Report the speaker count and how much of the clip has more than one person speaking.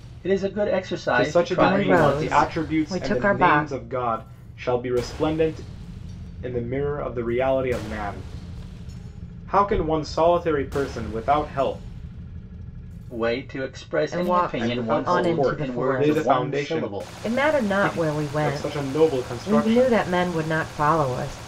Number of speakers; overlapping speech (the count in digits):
3, about 38%